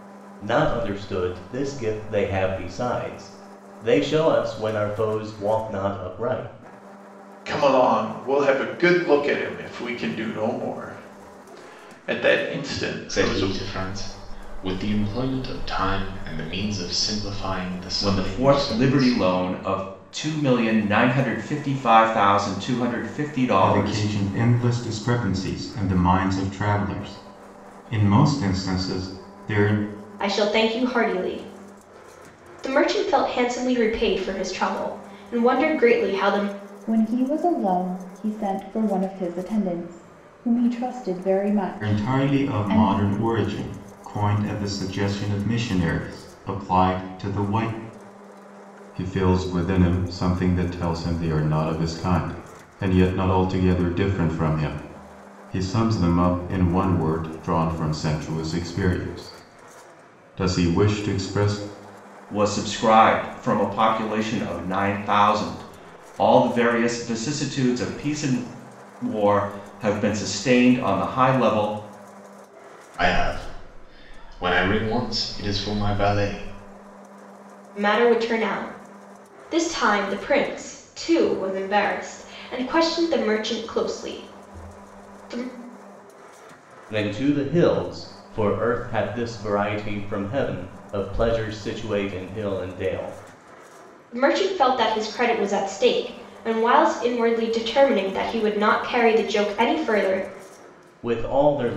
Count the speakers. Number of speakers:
7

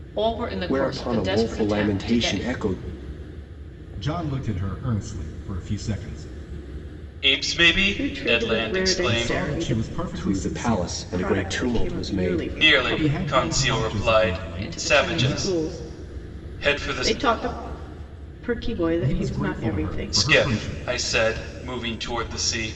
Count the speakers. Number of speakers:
5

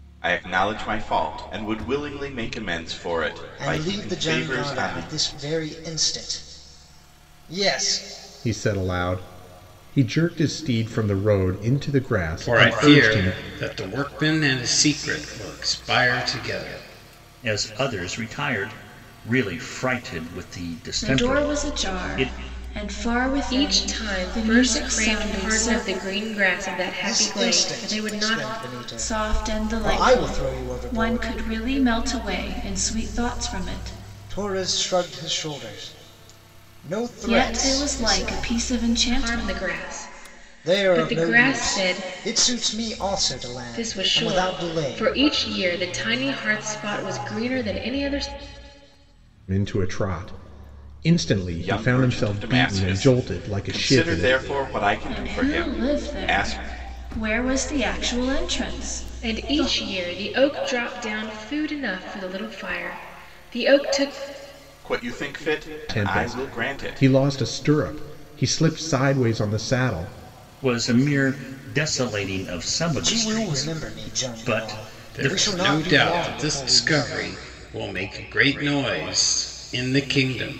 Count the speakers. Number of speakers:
7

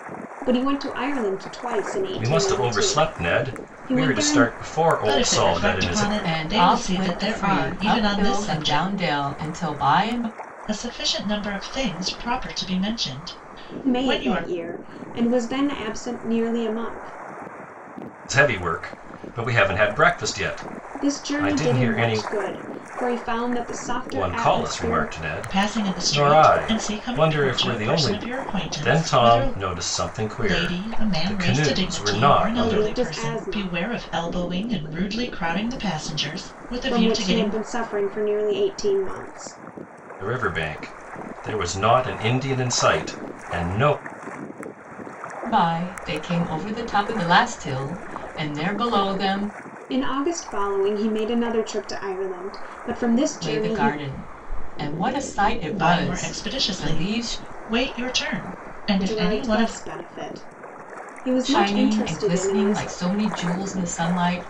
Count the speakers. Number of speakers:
4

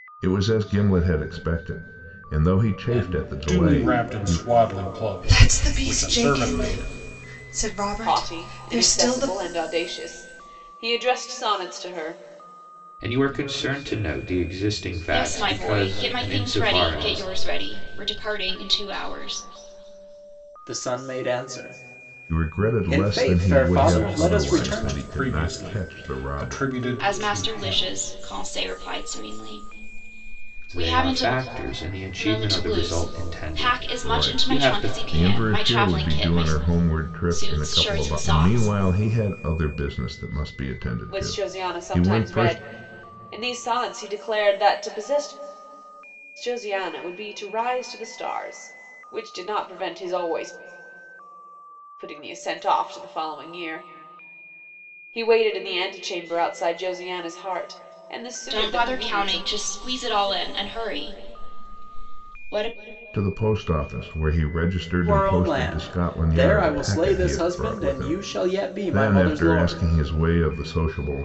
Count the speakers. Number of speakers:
7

